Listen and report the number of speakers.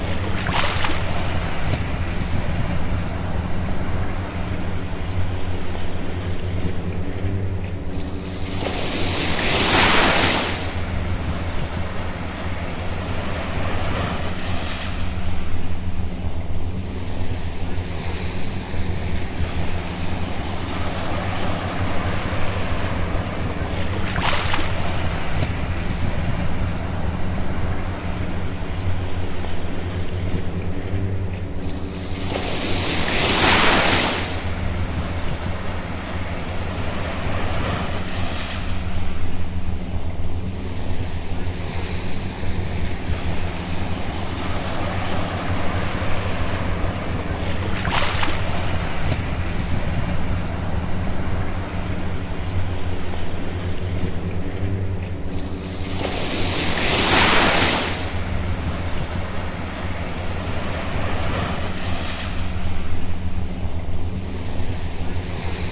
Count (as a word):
zero